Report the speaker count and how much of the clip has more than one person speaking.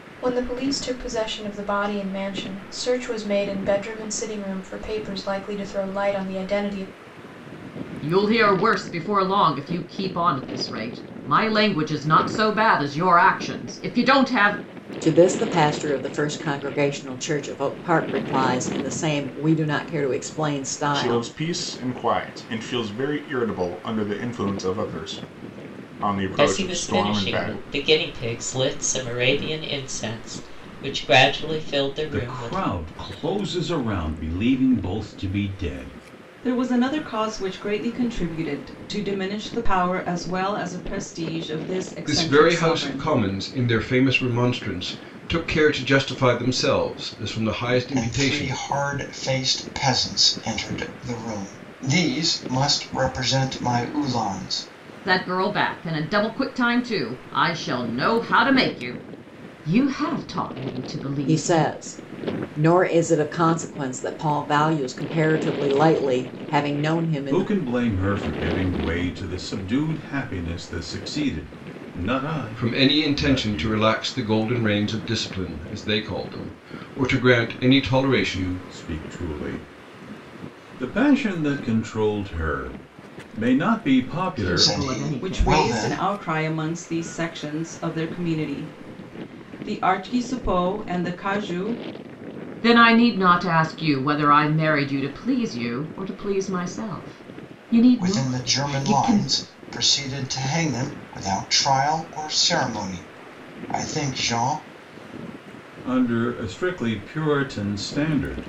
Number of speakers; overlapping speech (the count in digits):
9, about 9%